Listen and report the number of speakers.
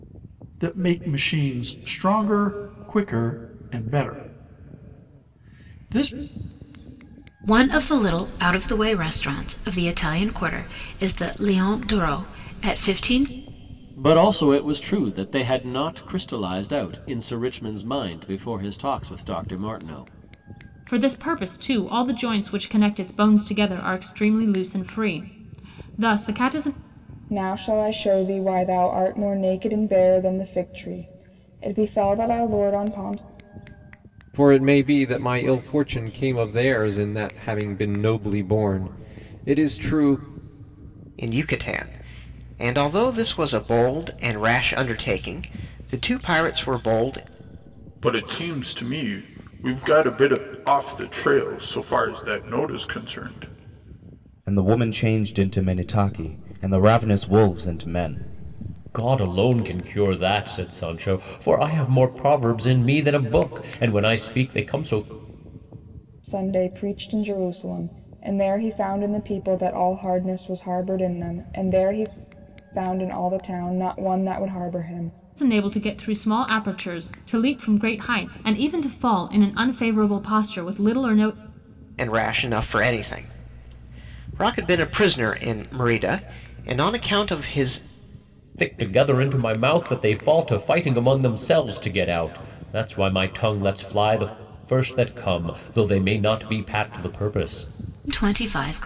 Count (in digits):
10